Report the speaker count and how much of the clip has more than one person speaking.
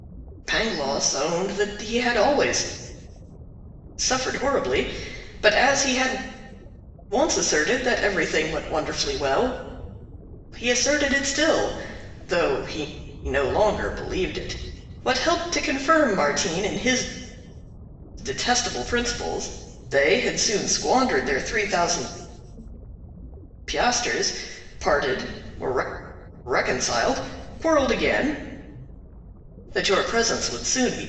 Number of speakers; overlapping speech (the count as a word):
one, no overlap